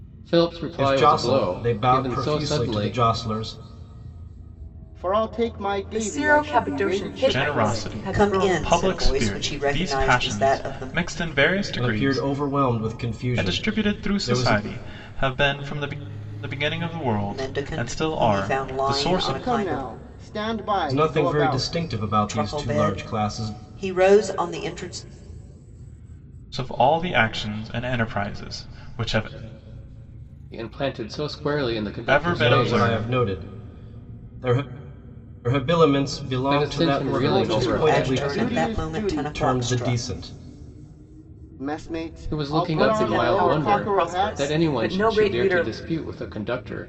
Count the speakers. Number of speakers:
six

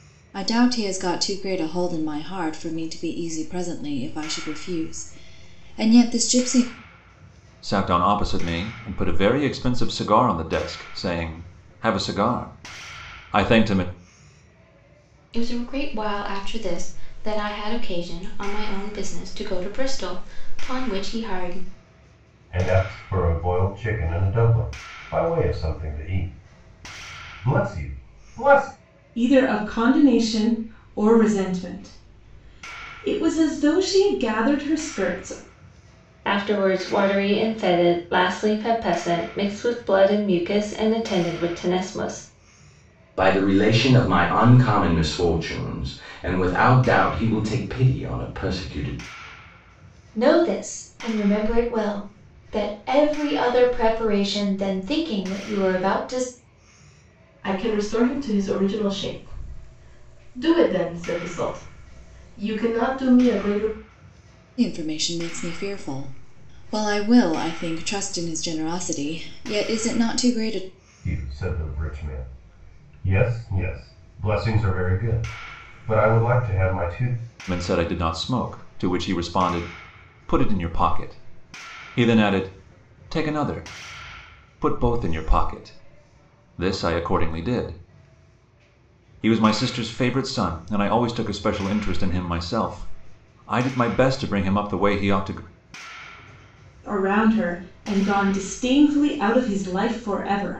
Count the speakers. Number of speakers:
nine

